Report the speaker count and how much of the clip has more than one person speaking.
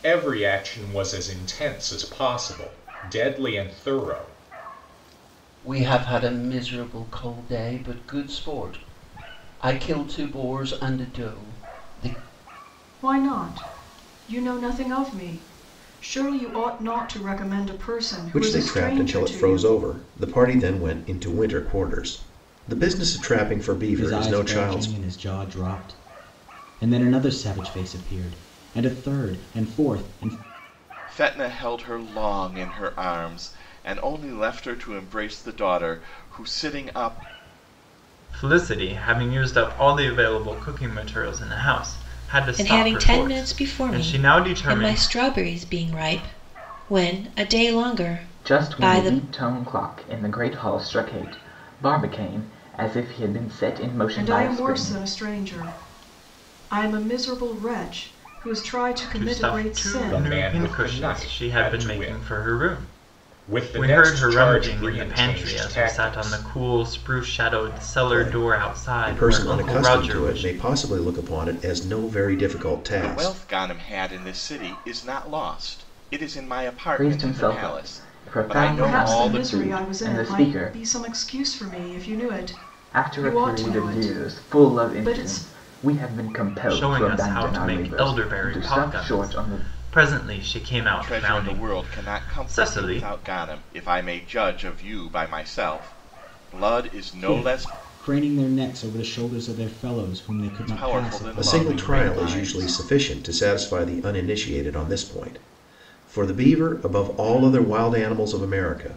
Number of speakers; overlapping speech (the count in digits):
9, about 28%